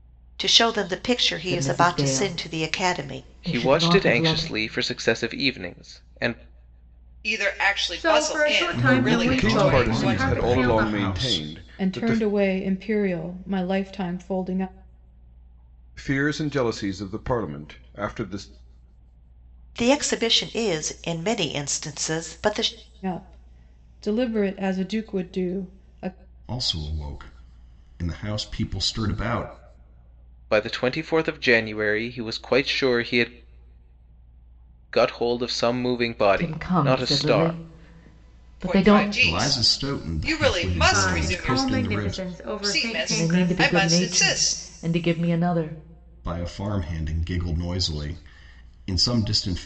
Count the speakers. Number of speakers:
8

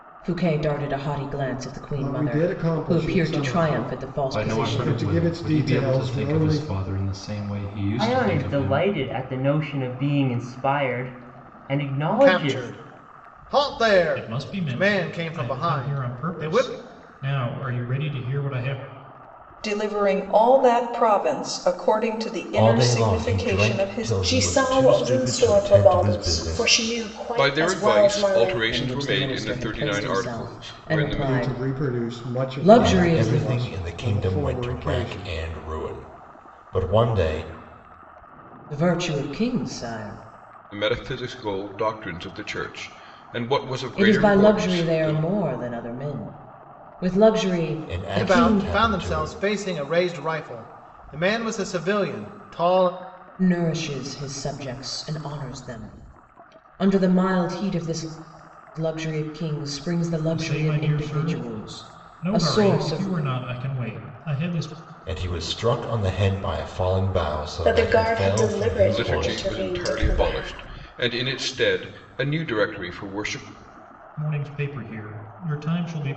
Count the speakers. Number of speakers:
10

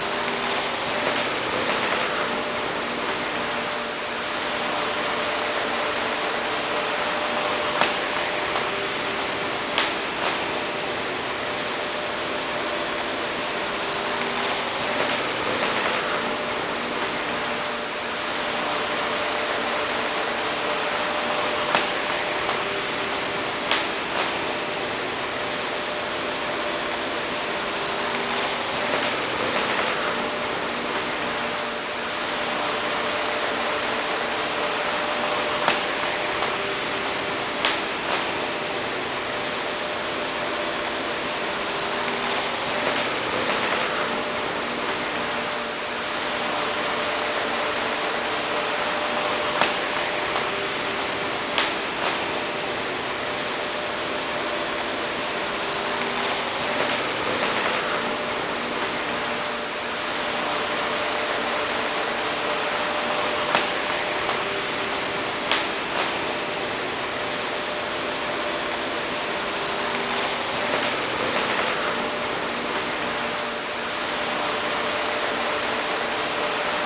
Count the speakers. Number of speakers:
0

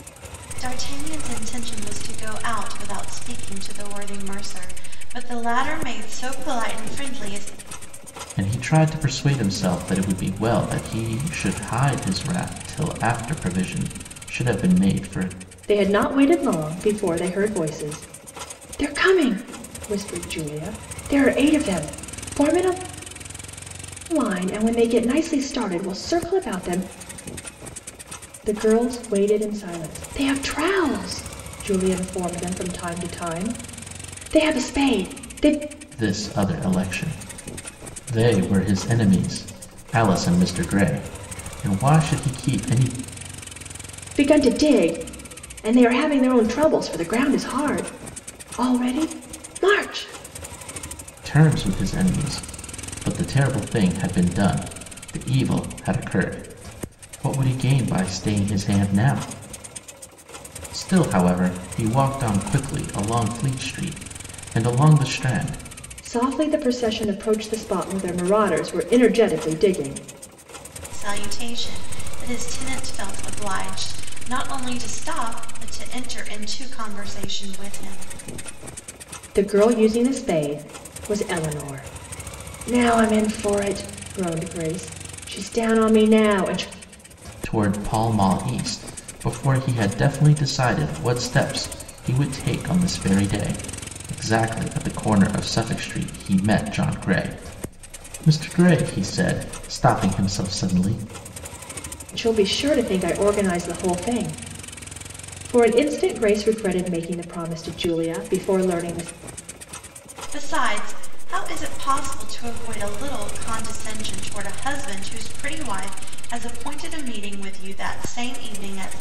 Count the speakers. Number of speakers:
3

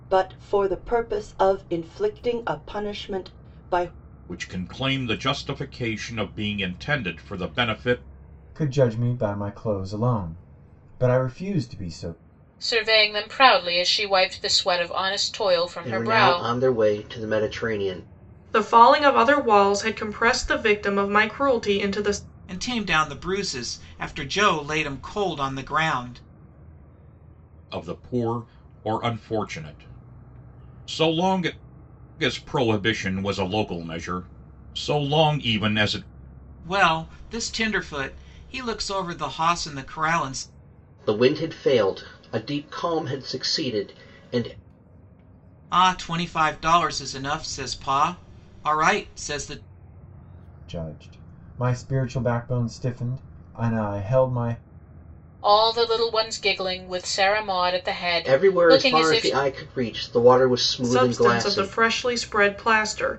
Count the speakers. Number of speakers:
7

